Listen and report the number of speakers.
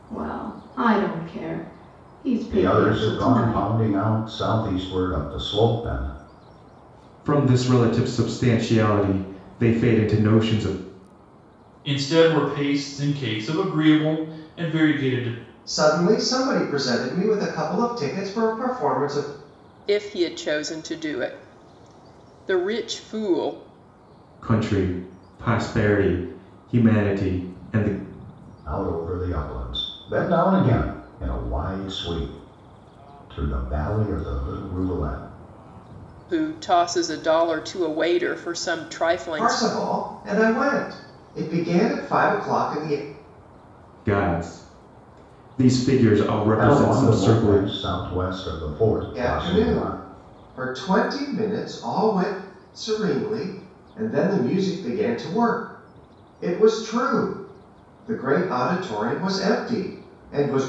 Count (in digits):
6